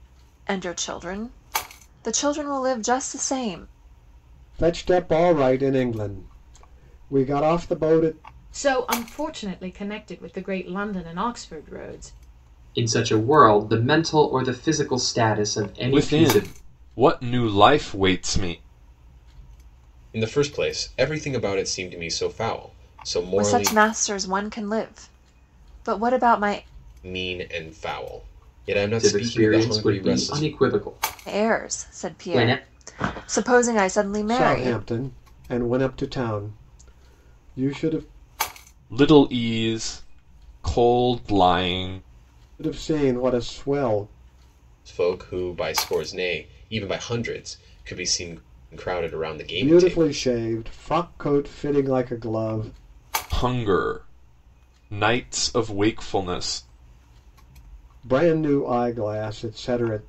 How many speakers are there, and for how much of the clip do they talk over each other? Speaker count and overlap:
6, about 9%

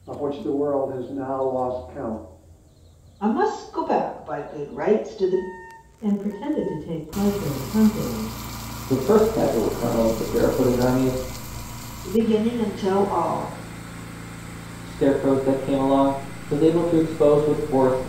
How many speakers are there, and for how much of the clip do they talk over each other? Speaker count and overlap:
4, no overlap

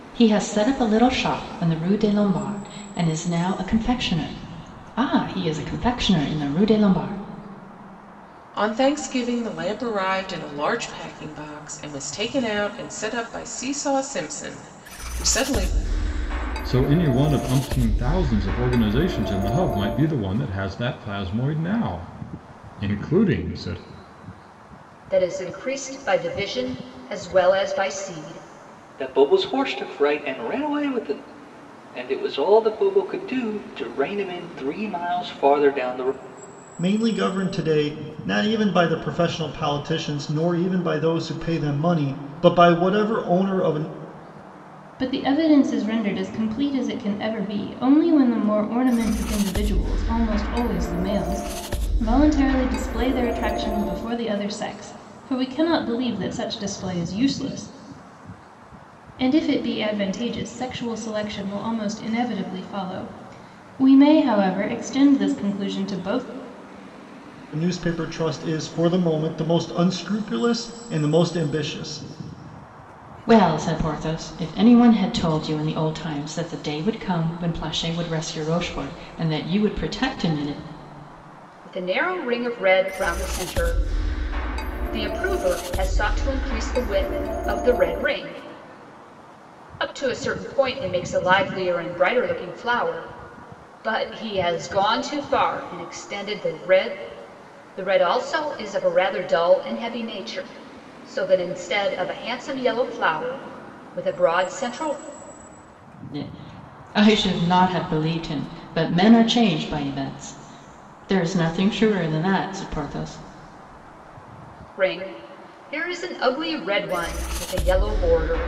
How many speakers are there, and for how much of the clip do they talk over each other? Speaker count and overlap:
7, no overlap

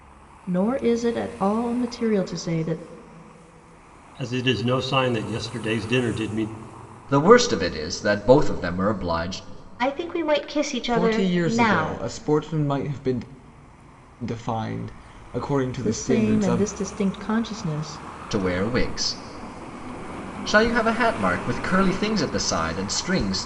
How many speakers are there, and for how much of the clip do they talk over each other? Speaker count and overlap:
5, about 9%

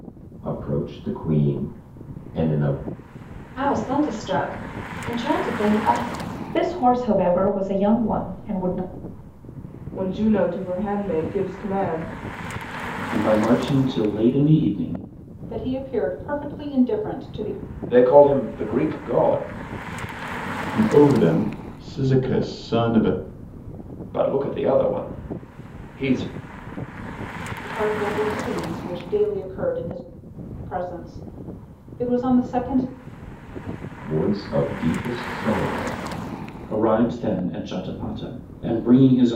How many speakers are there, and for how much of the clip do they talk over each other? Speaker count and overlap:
8, no overlap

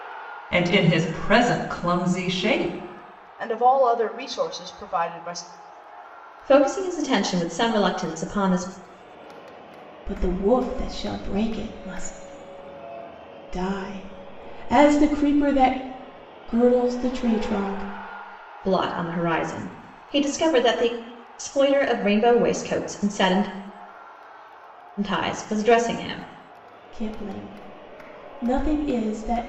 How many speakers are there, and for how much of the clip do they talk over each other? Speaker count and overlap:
4, no overlap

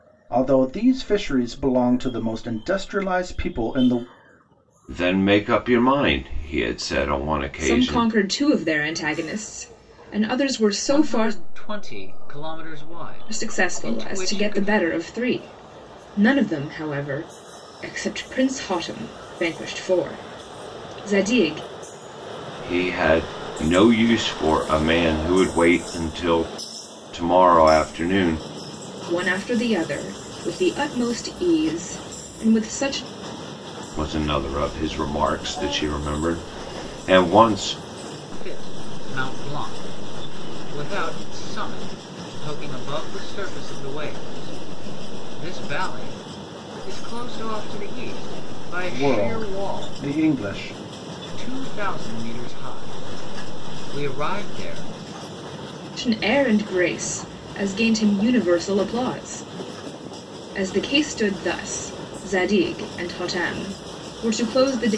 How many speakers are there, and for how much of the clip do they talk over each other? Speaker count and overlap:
4, about 5%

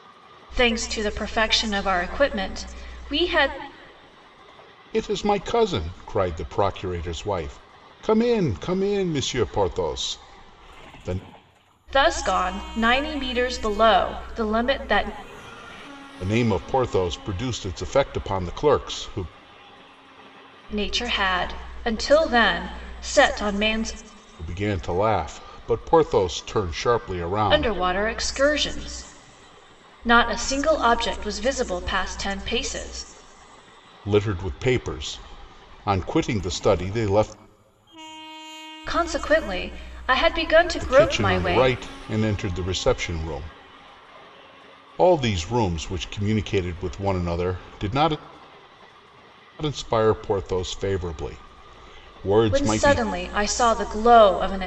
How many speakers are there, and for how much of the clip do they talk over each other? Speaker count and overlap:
2, about 3%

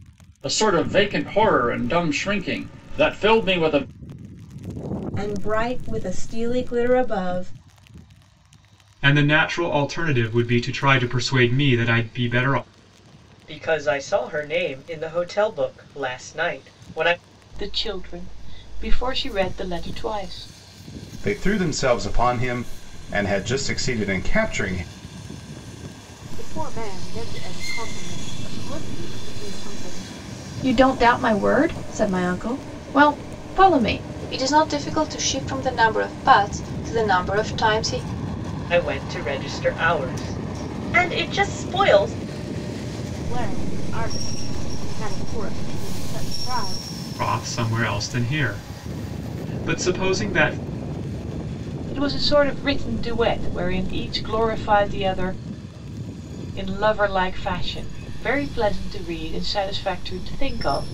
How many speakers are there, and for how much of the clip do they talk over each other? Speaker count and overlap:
9, no overlap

